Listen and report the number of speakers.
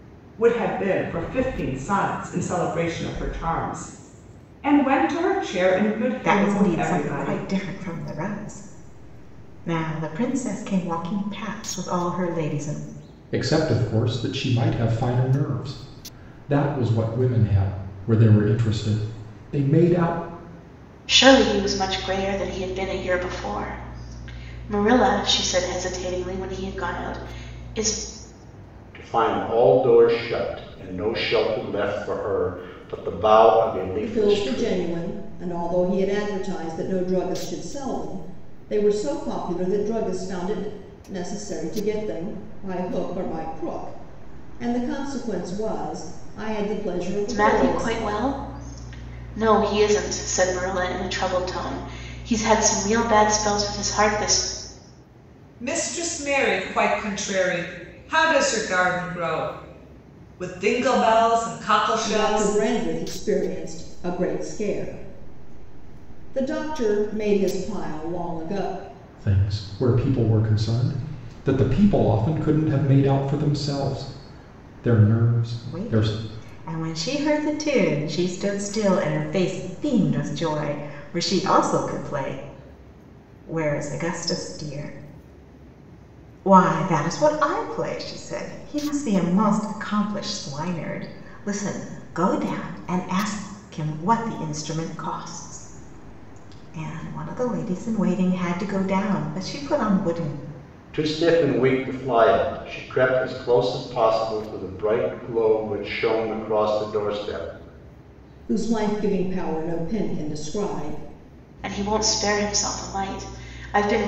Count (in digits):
6